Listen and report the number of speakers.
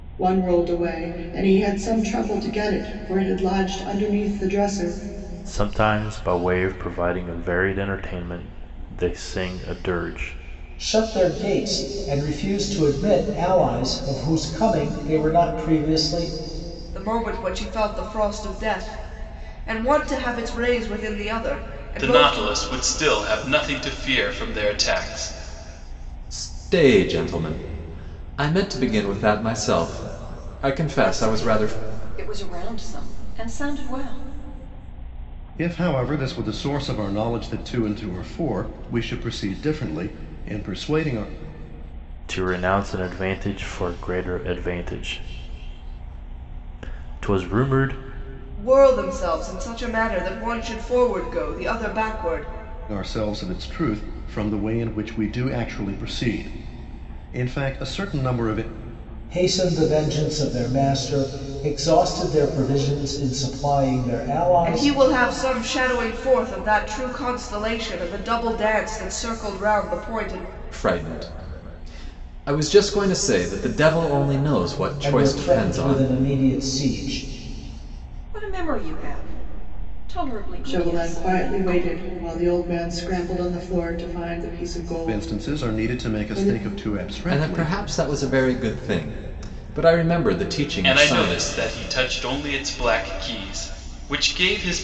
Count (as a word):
eight